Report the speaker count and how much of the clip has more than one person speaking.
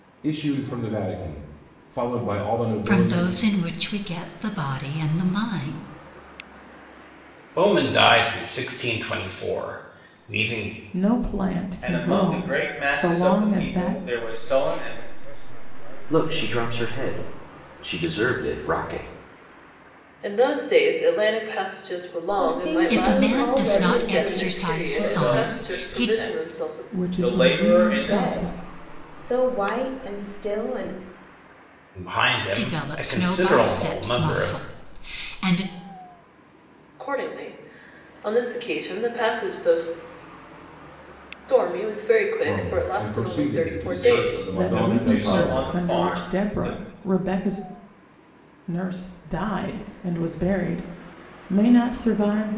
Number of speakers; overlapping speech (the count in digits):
9, about 34%